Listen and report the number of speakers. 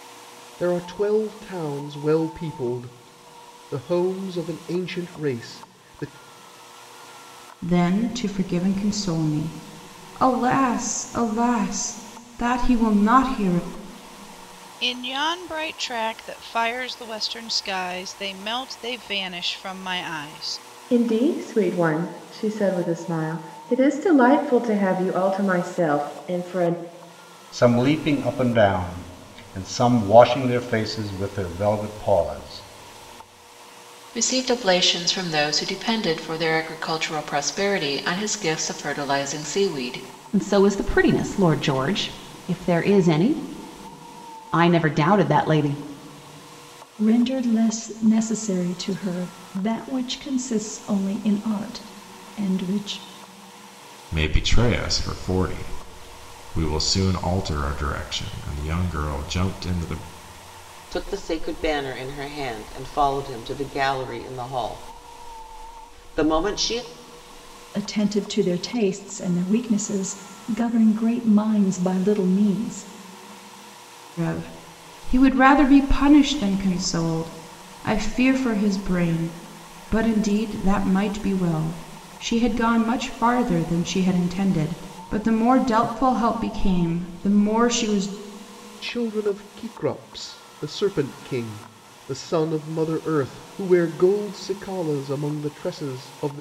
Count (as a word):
ten